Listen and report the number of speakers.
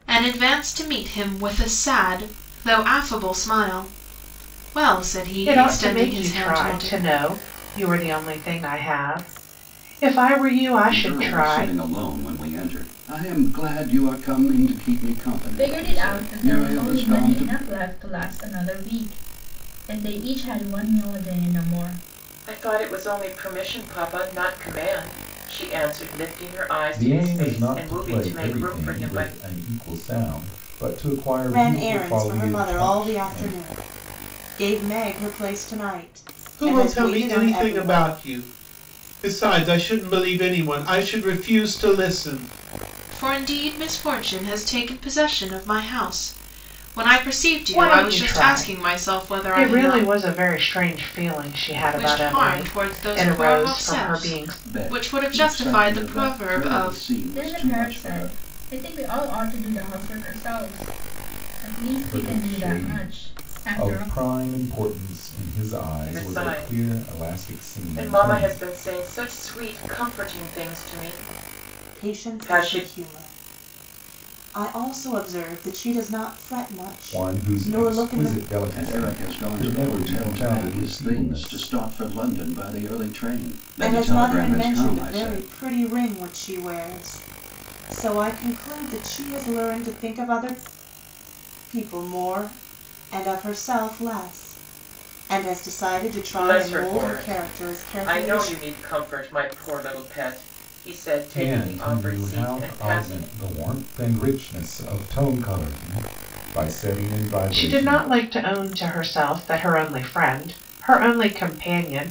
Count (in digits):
8